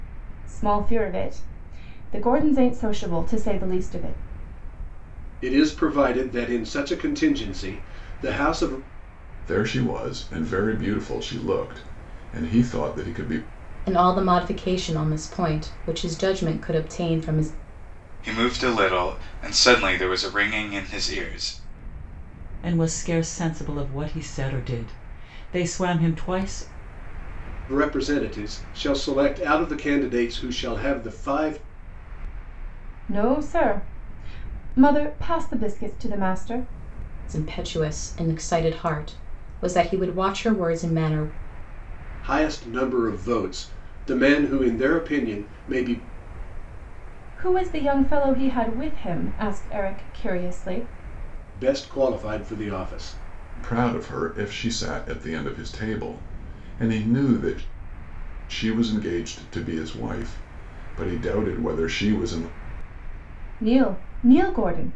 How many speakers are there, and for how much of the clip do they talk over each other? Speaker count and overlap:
6, no overlap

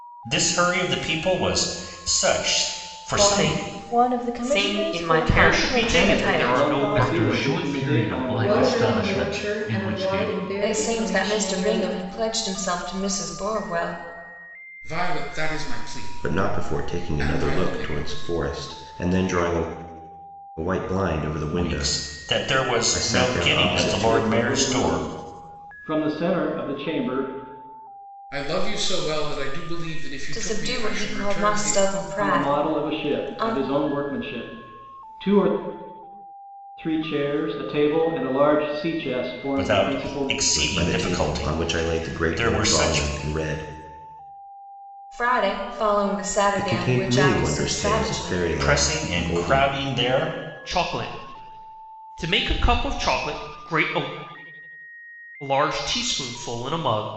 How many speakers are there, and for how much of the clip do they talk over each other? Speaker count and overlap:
10, about 41%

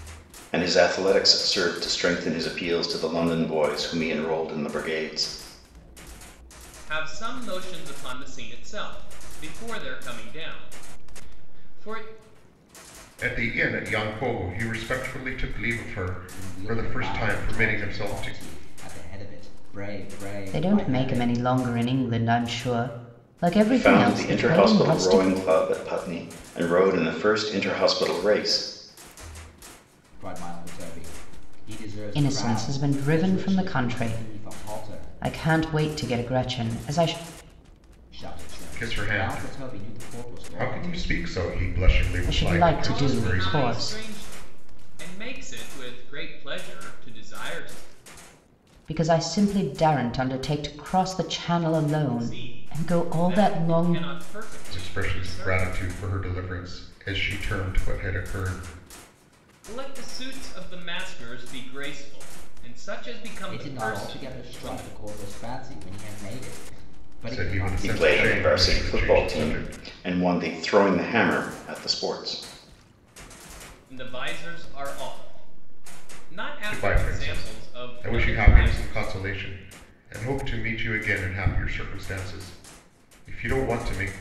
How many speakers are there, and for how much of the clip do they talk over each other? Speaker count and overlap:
5, about 25%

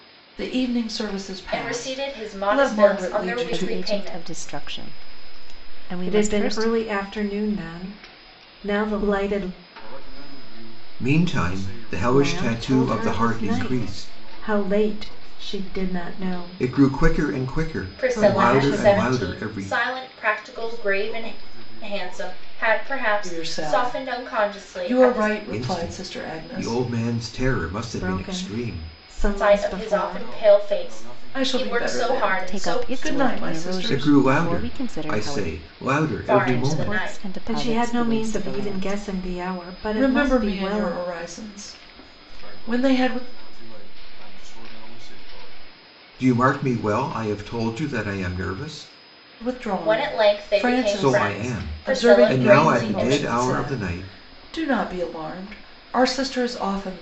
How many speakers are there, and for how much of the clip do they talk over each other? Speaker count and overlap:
6, about 60%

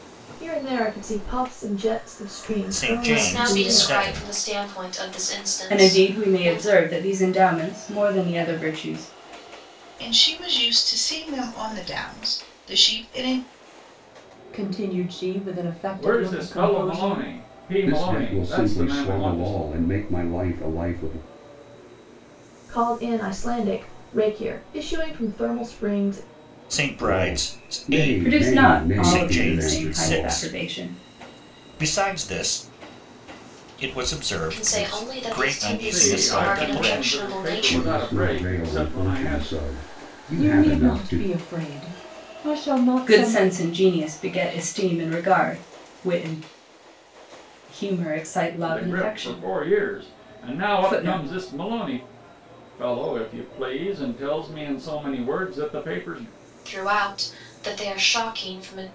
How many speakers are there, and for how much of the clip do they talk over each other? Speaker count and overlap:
8, about 32%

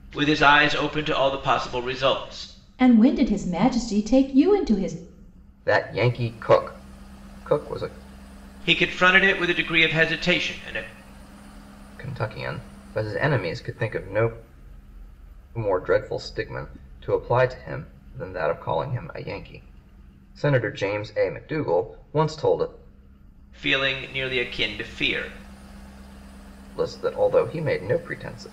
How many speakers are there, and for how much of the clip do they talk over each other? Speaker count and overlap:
3, no overlap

